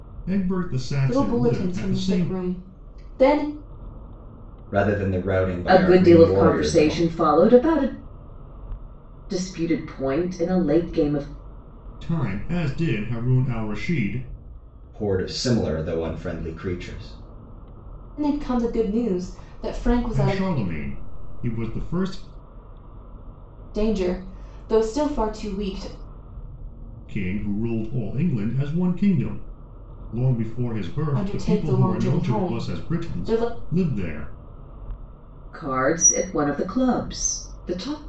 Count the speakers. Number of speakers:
four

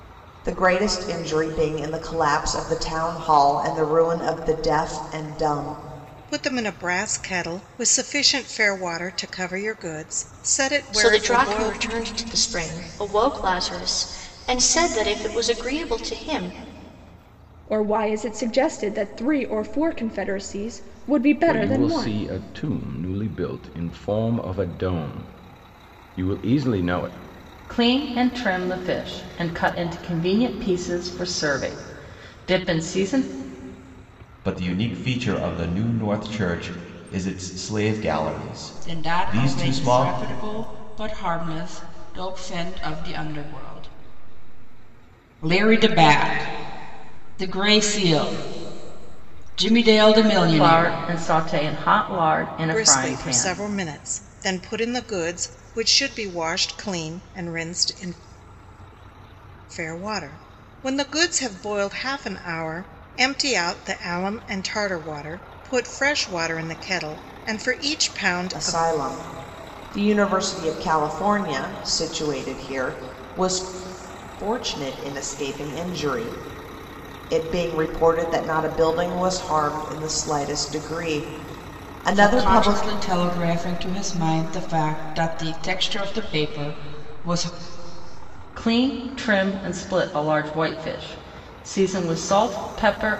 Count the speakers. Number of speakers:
eight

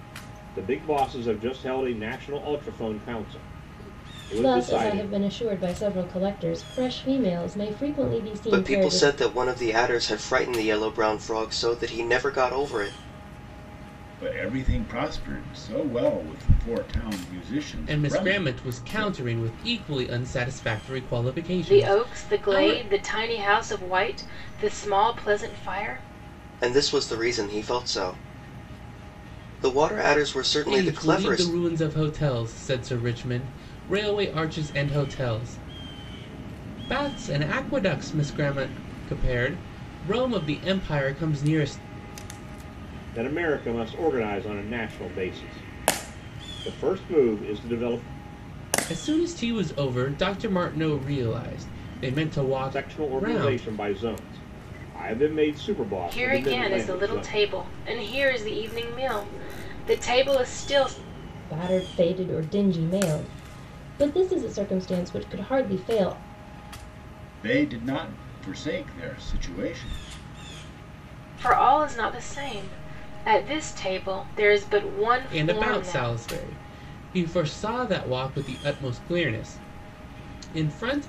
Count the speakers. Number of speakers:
six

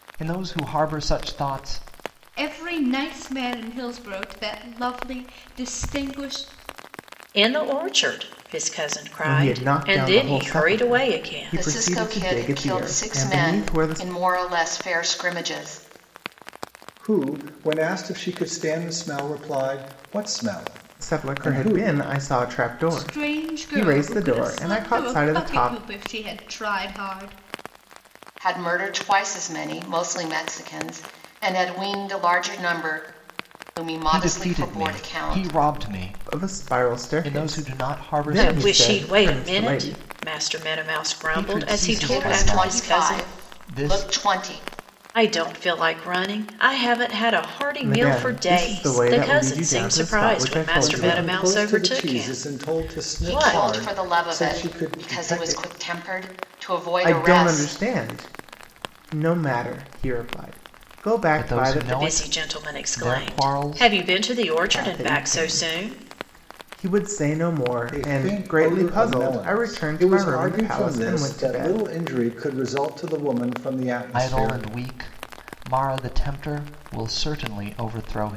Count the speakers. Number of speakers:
six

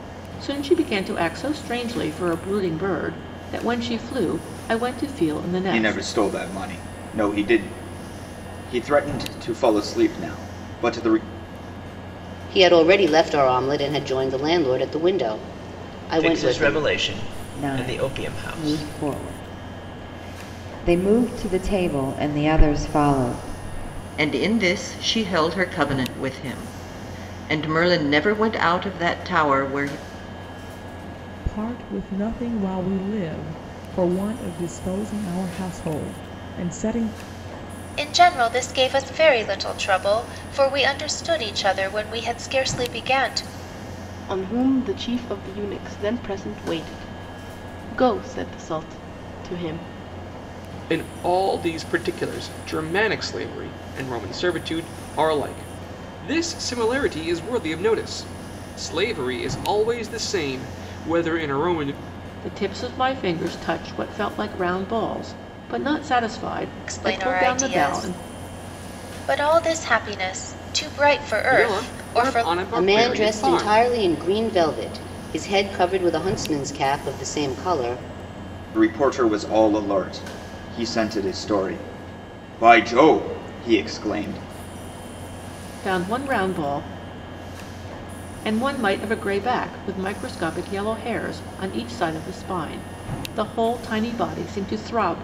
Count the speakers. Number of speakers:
ten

